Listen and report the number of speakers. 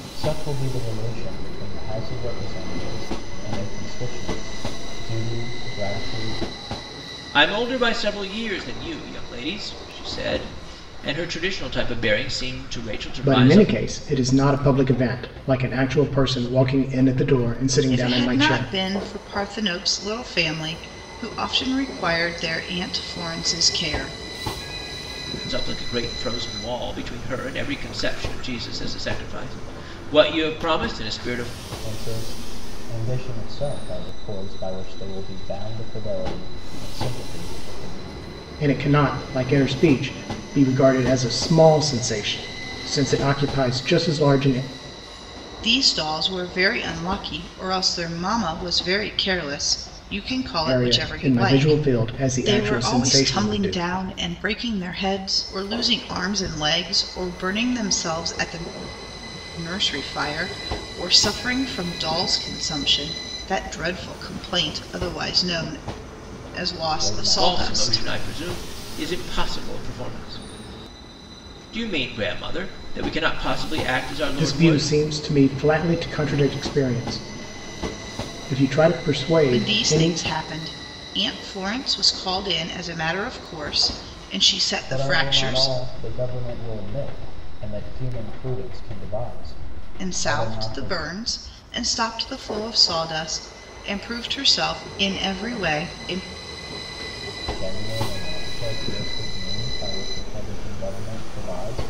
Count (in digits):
4